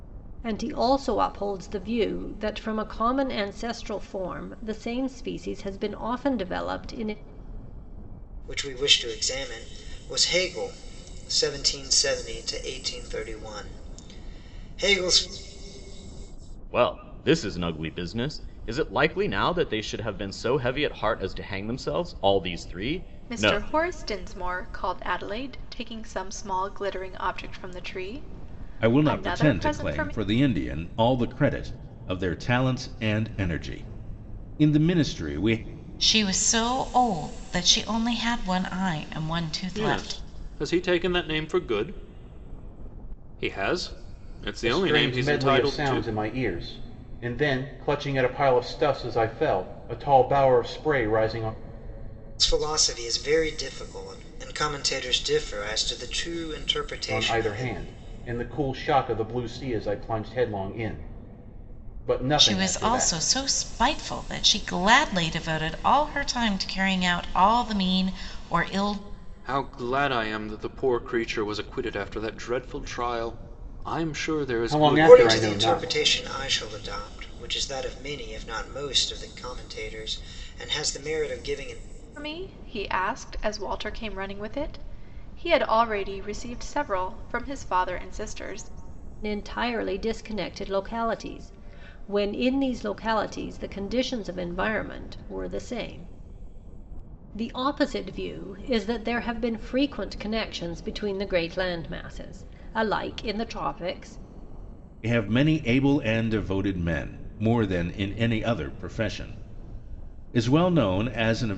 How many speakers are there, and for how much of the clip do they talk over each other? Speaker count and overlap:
eight, about 6%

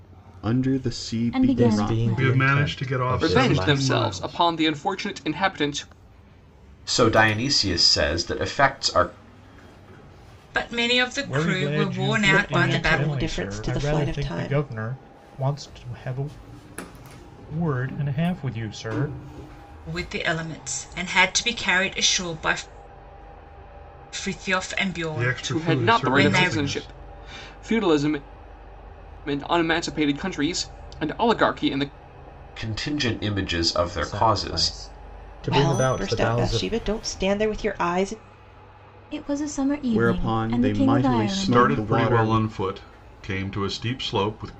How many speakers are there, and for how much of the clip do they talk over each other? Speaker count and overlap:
nine, about 29%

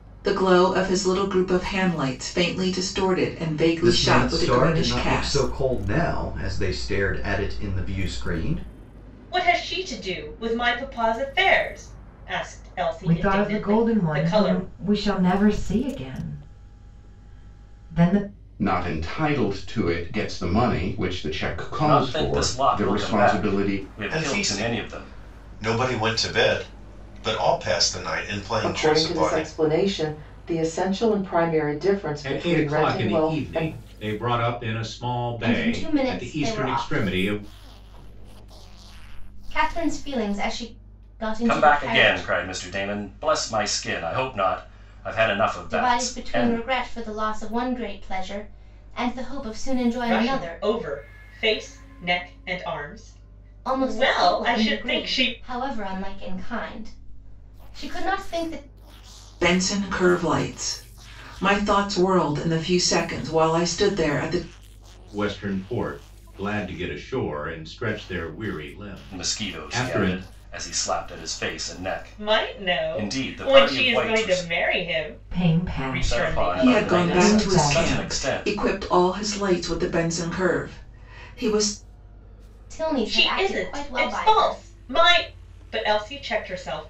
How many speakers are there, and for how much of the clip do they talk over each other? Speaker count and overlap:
ten, about 27%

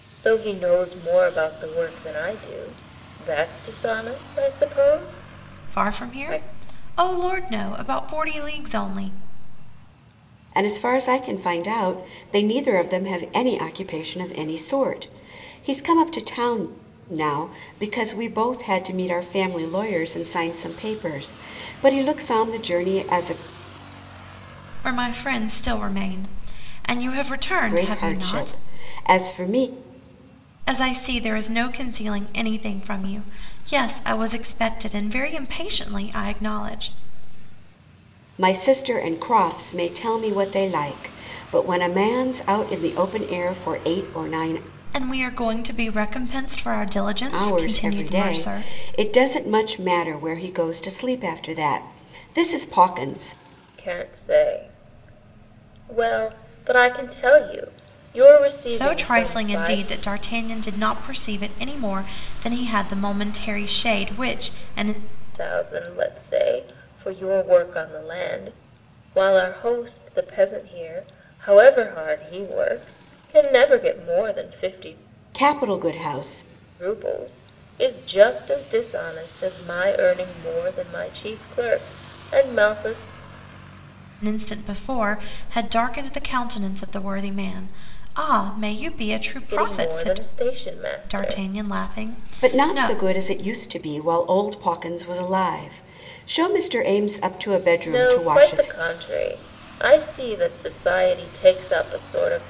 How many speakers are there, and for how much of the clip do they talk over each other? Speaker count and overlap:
three, about 7%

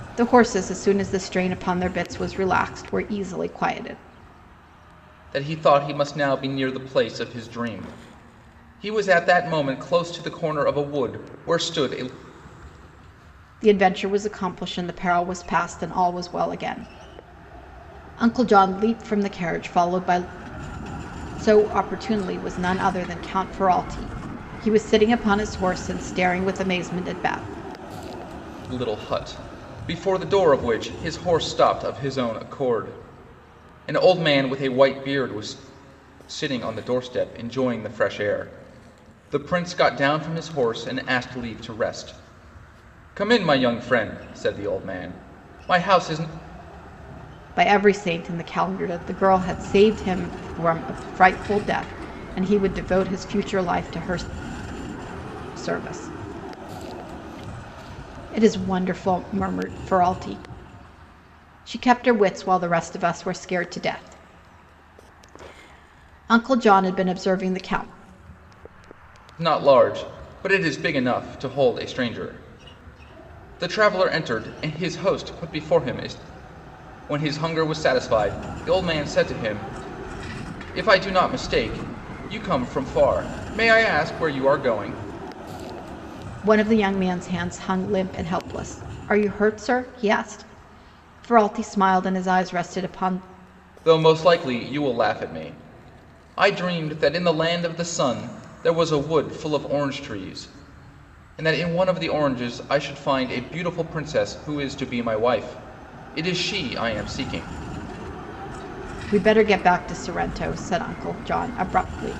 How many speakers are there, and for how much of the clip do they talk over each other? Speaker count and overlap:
two, no overlap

